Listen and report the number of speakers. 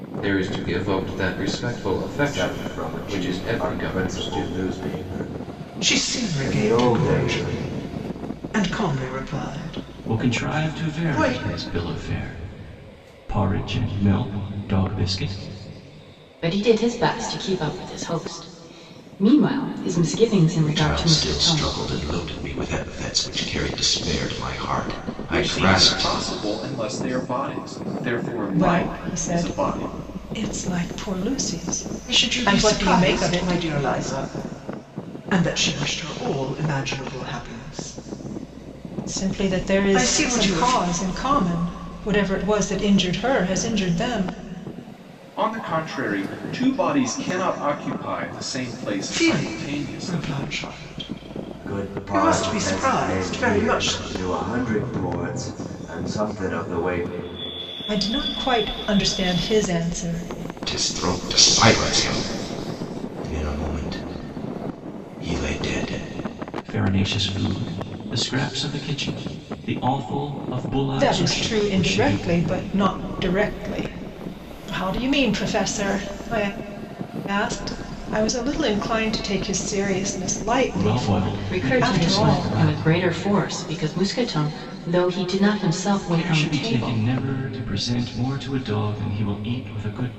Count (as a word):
eight